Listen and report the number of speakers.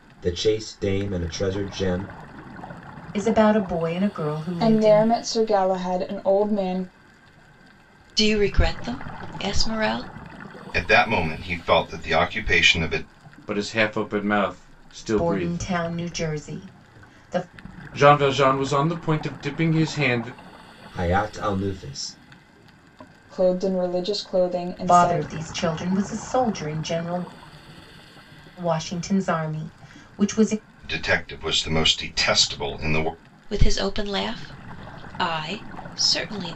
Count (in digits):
6